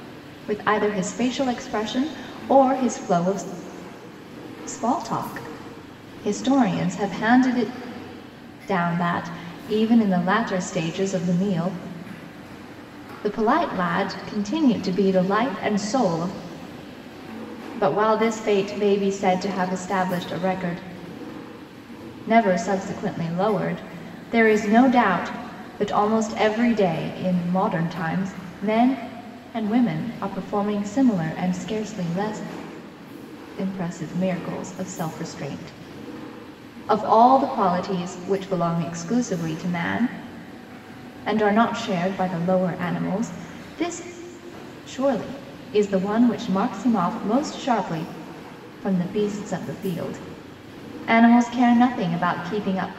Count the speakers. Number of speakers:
one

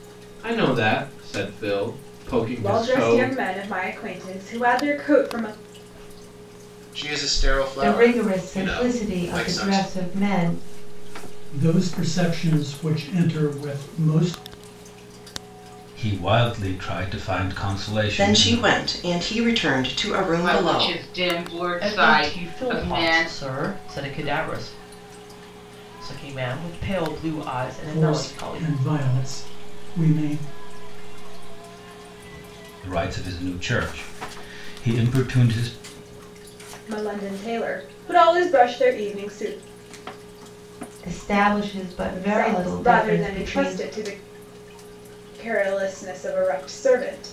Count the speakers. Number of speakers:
ten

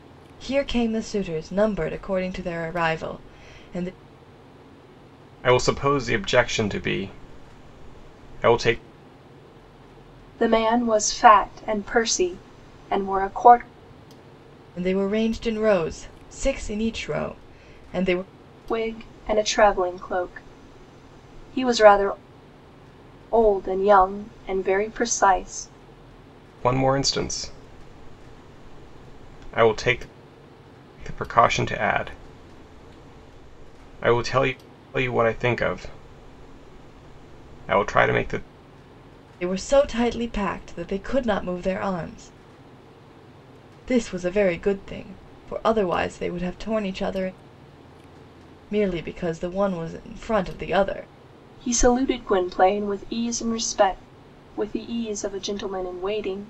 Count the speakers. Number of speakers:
three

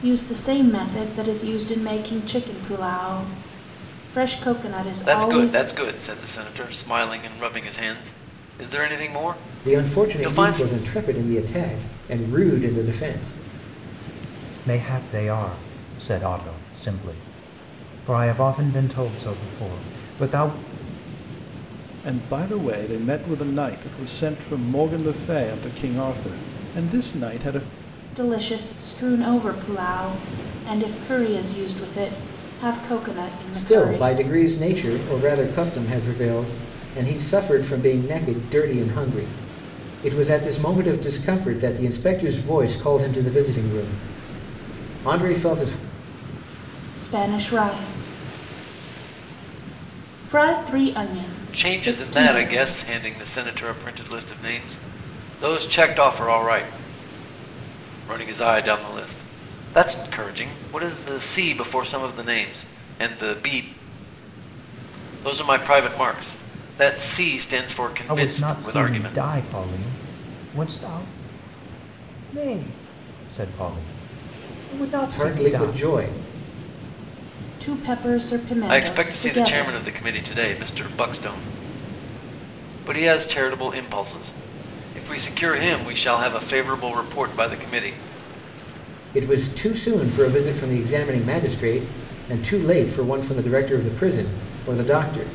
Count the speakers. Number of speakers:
five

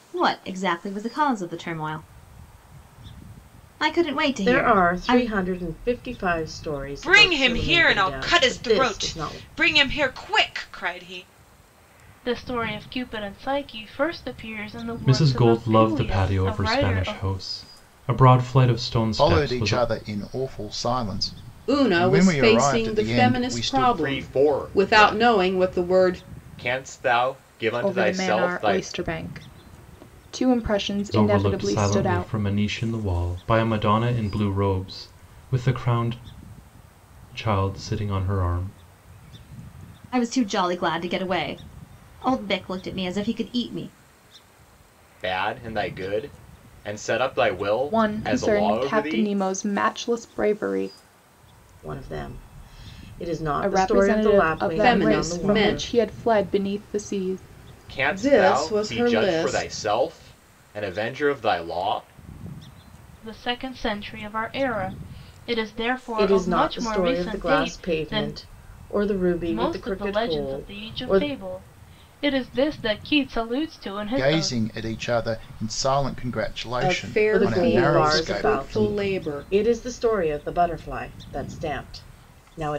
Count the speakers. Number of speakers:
nine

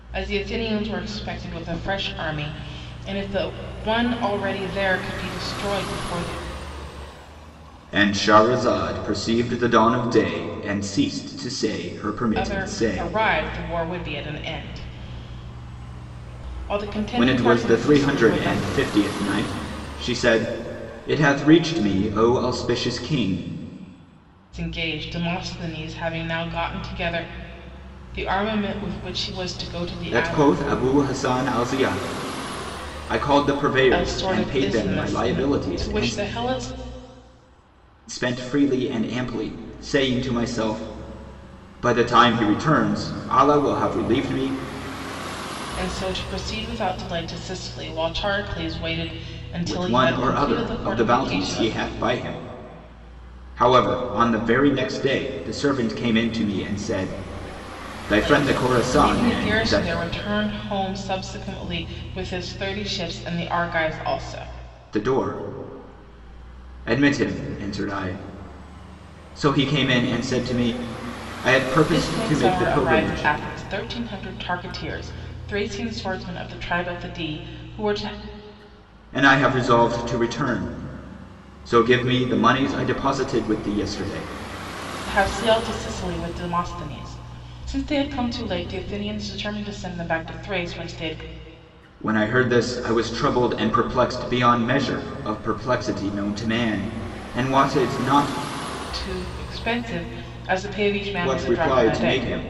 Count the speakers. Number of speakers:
two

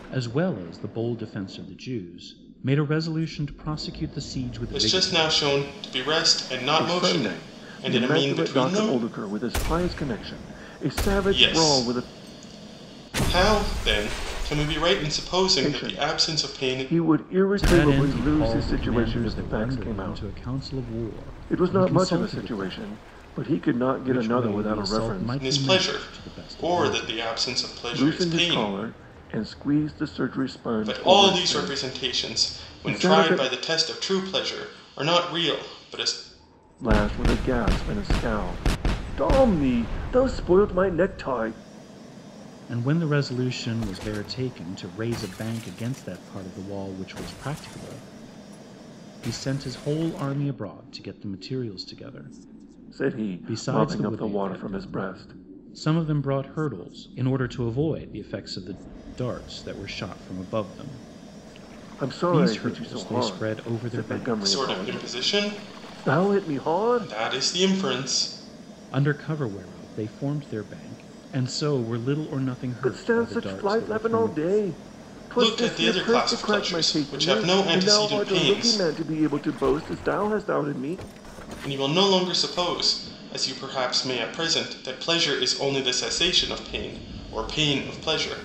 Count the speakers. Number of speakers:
three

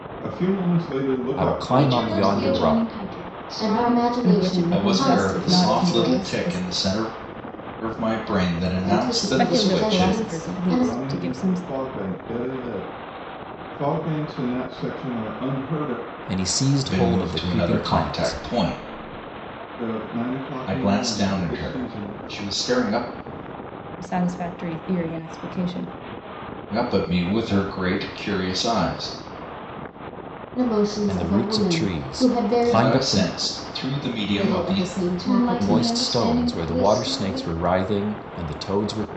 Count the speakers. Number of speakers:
six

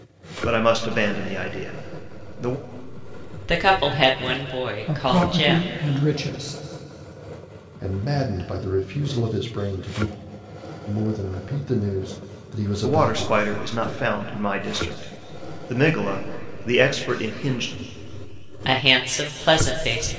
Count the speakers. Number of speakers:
four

